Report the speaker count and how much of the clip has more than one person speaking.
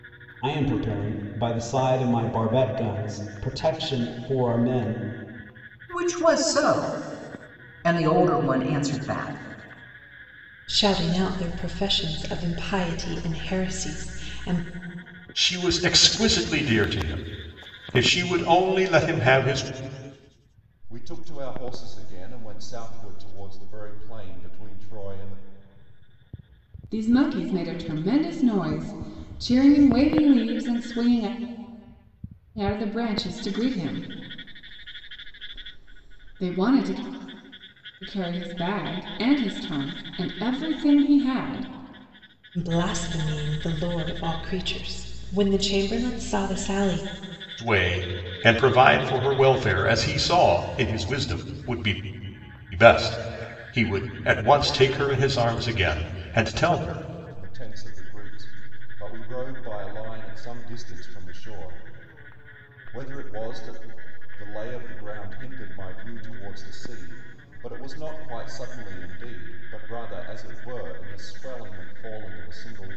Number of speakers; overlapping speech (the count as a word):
six, no overlap